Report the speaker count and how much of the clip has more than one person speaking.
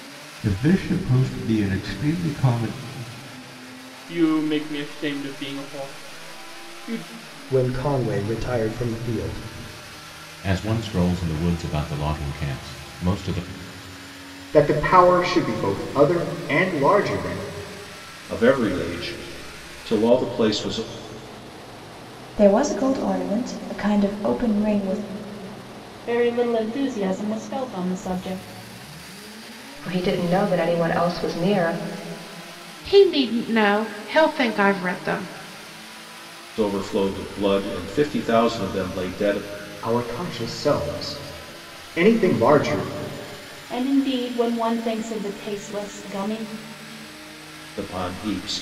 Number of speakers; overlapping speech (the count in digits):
10, no overlap